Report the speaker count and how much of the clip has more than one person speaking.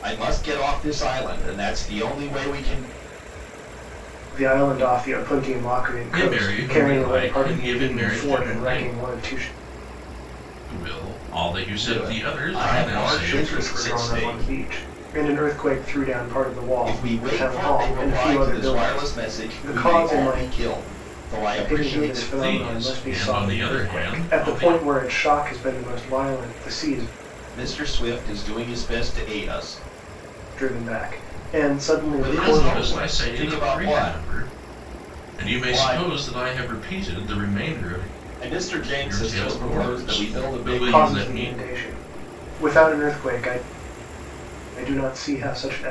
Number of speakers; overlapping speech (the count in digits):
3, about 39%